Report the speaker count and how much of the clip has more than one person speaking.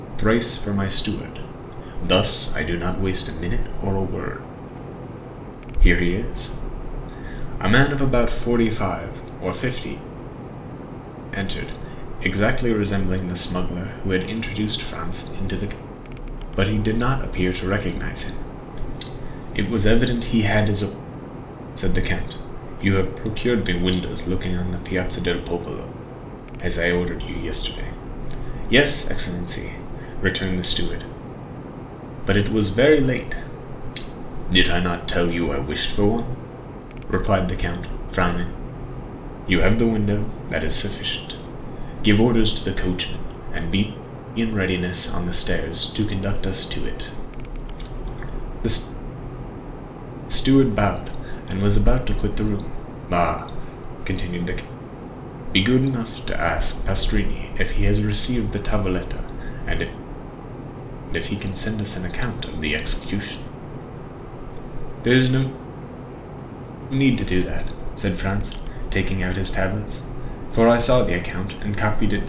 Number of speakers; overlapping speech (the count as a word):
one, no overlap